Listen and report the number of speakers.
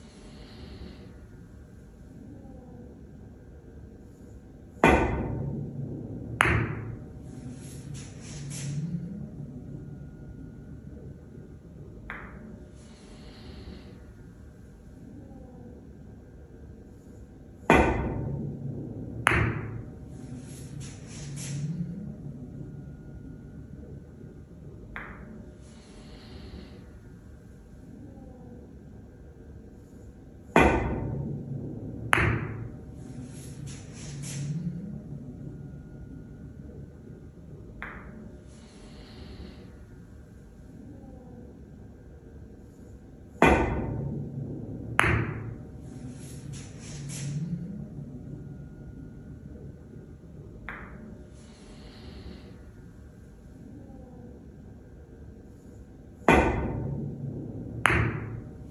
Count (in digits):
0